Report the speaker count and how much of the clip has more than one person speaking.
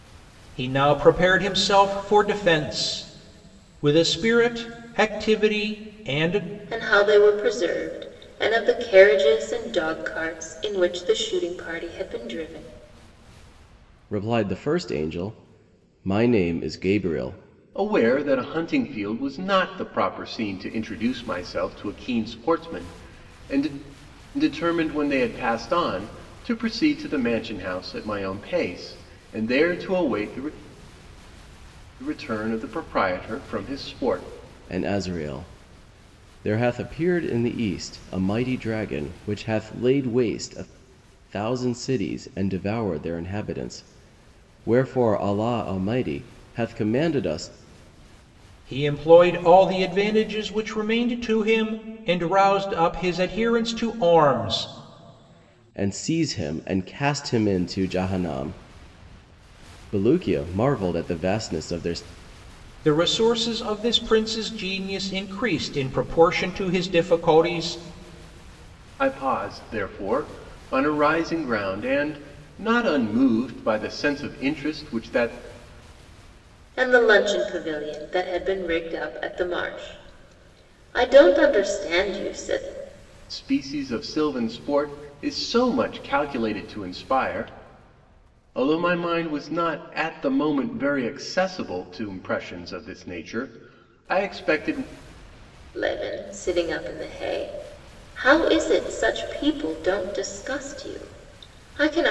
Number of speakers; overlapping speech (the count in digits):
4, no overlap